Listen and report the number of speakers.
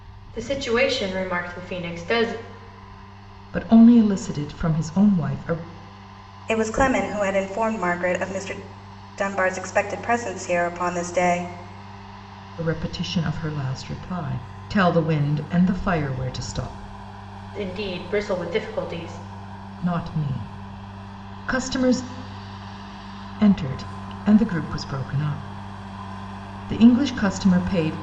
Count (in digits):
3